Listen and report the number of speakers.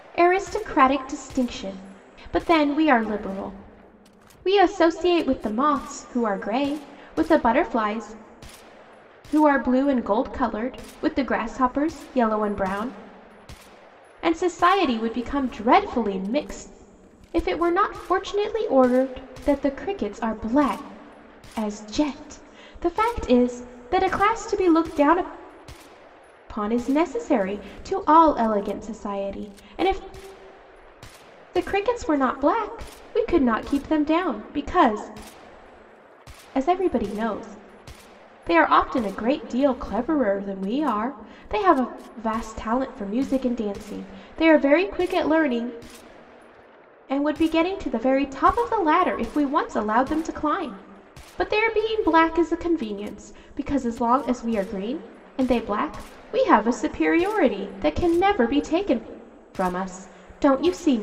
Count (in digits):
1